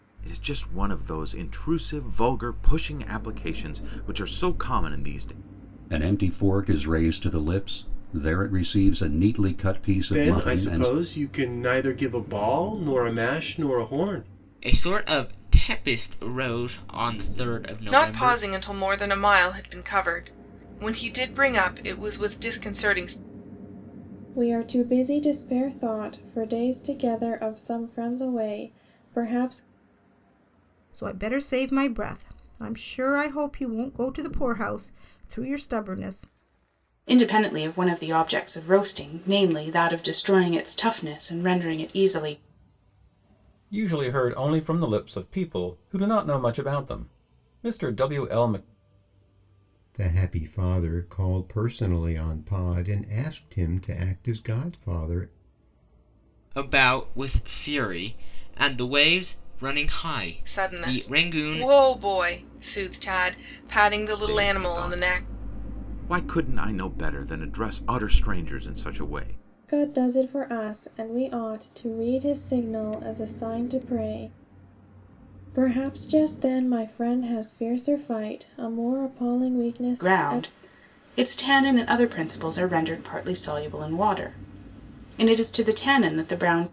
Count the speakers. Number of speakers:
10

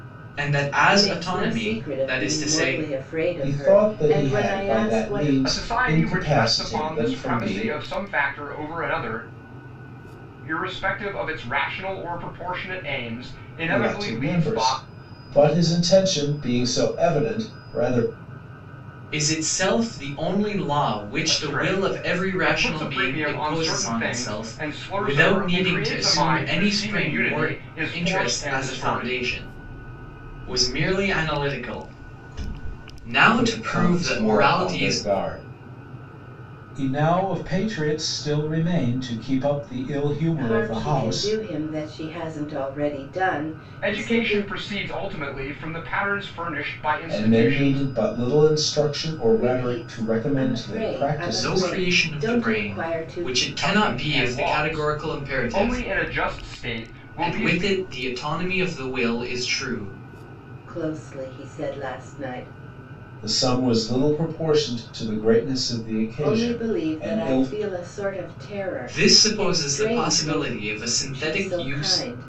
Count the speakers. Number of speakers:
4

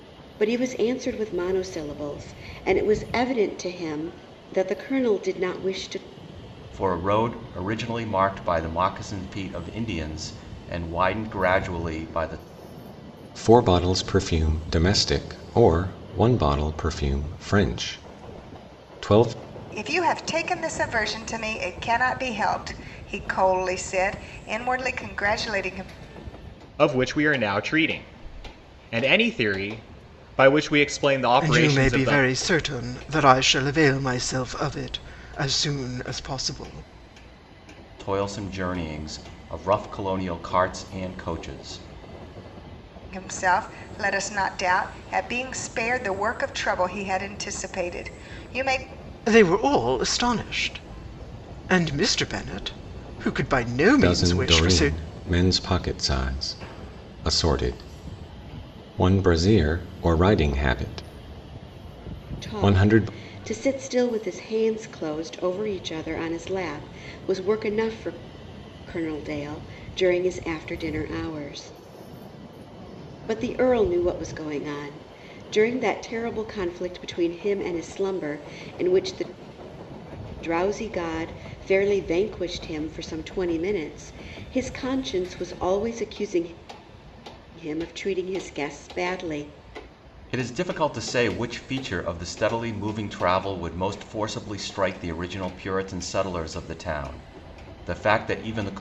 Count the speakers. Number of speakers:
6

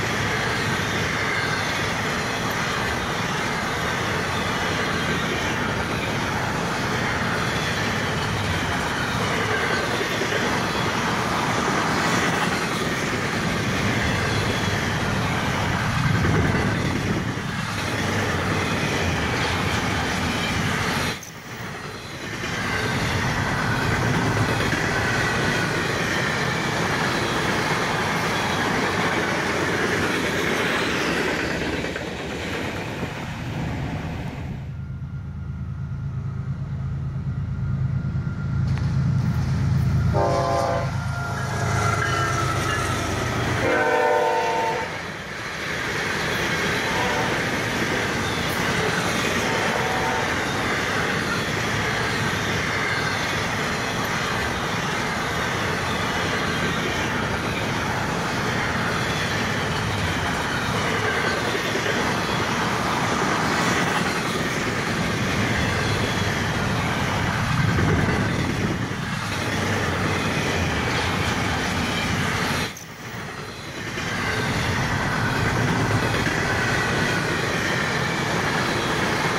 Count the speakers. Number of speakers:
0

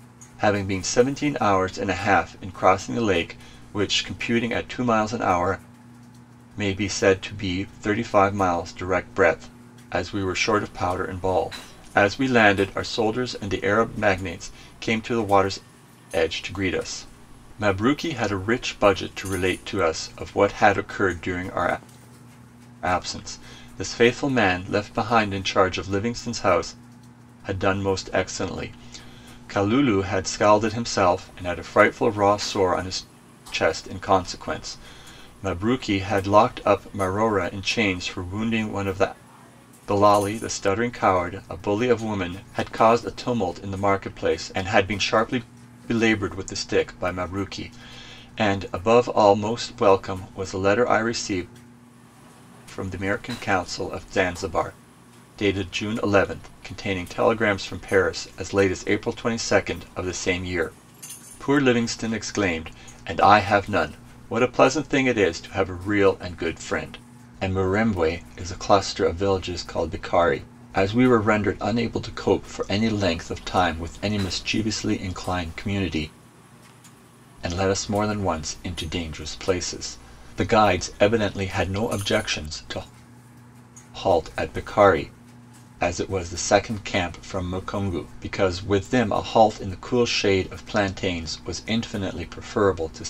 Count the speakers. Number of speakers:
1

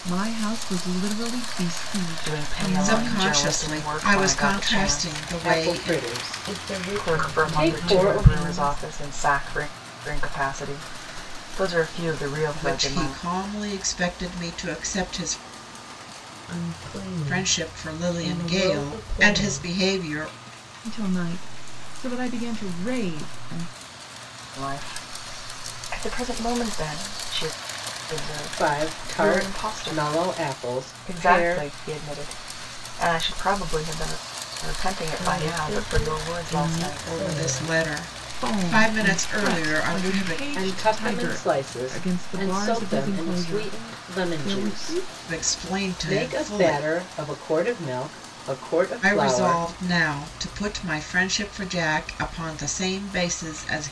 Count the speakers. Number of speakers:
5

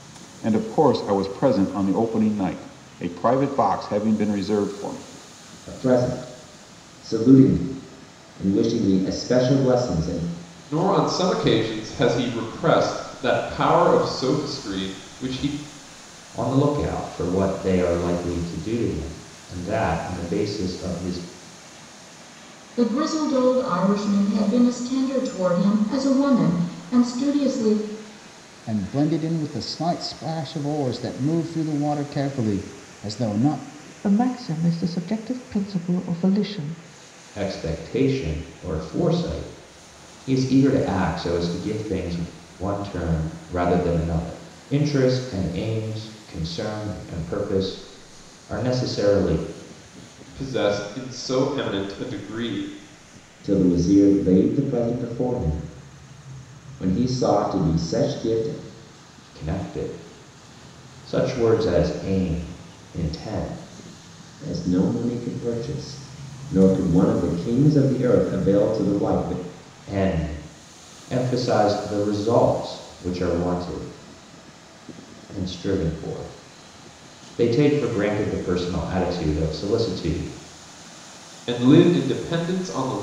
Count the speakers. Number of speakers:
7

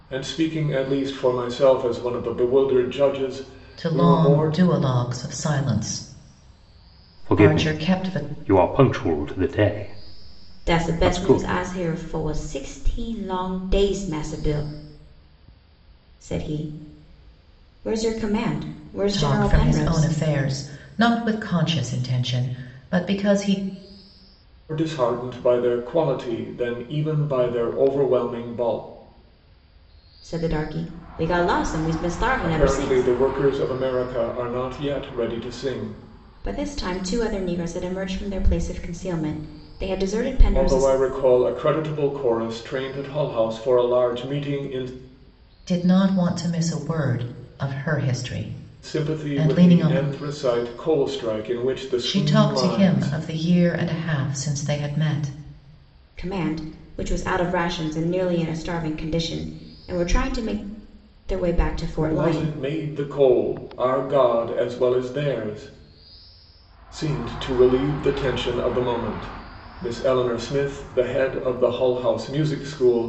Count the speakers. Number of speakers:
4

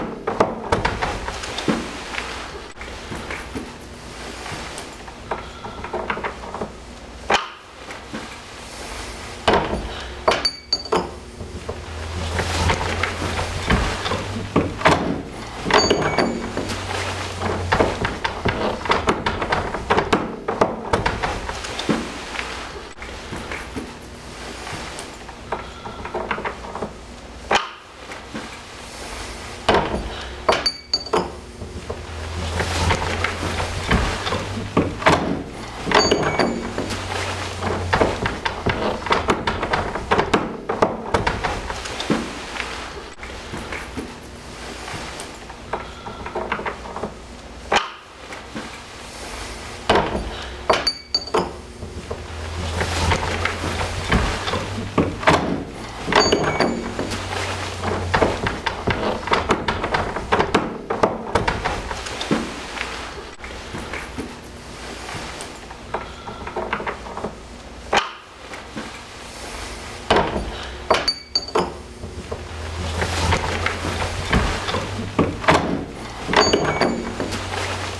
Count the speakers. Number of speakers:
0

